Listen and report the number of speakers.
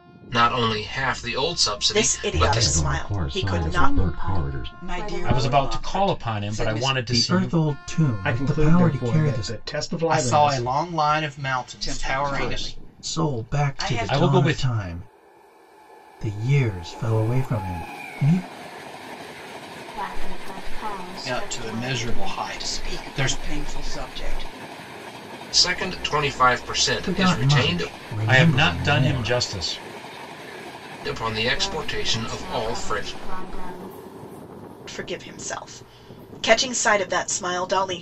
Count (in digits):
9